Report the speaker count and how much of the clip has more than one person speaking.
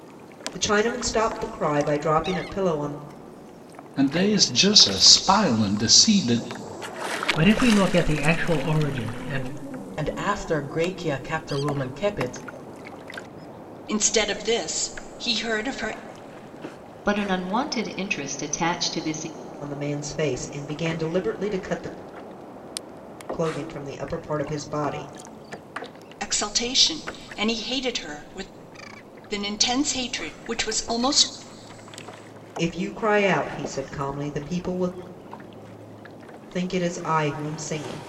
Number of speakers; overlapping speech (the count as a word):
six, no overlap